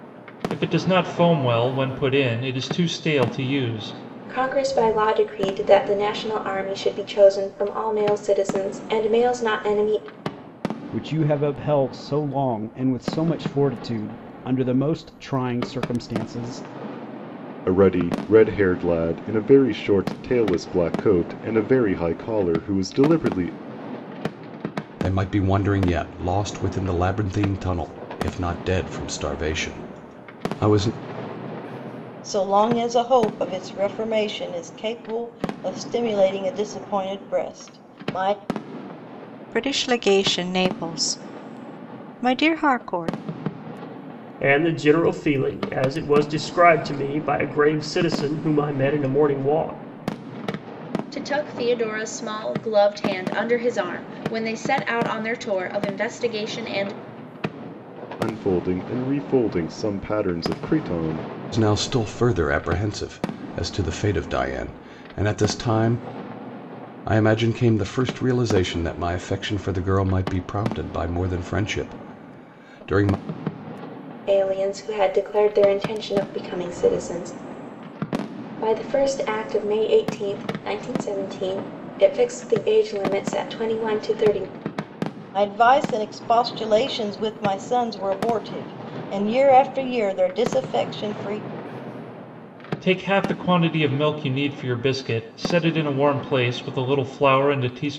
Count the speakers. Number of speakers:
9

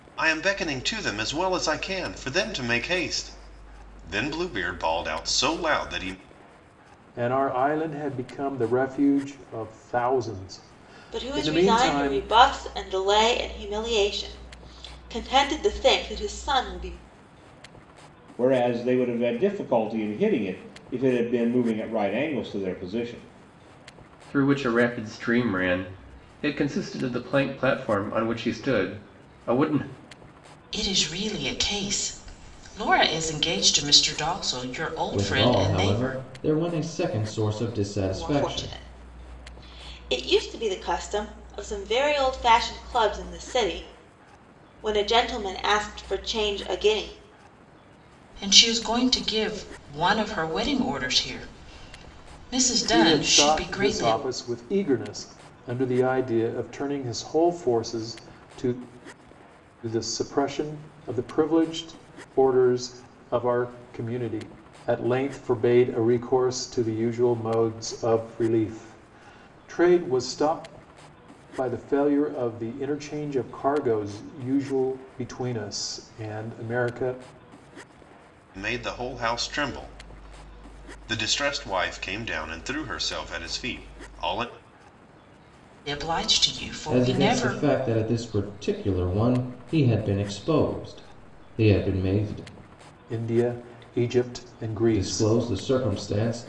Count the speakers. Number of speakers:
7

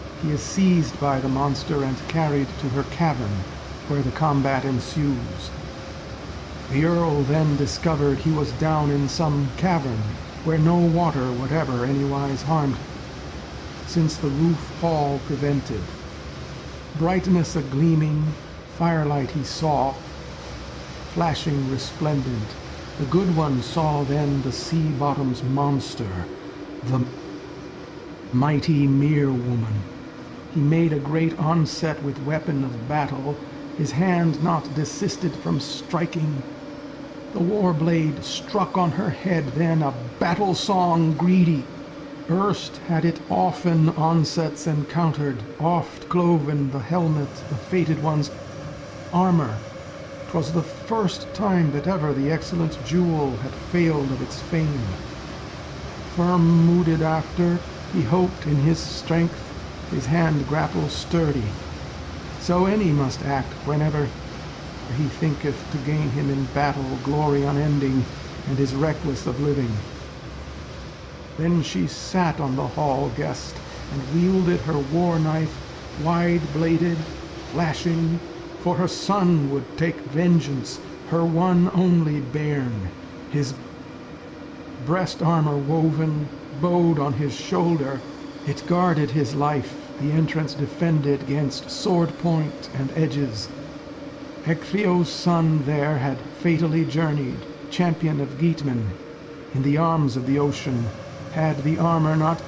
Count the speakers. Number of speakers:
1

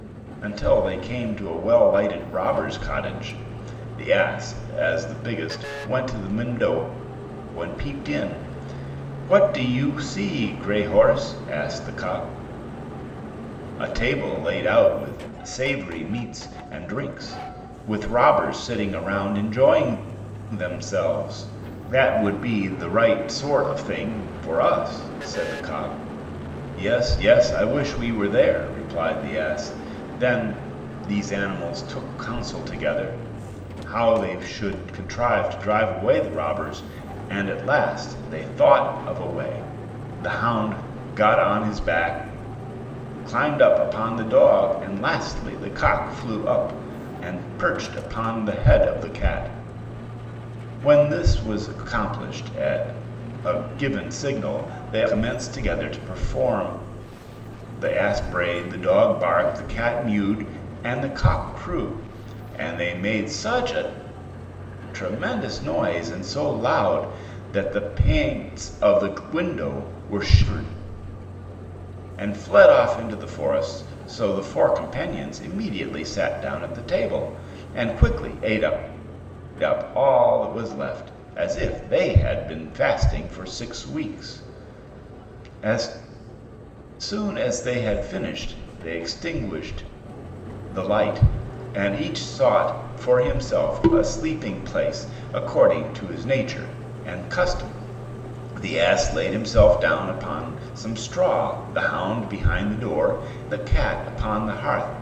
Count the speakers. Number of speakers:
1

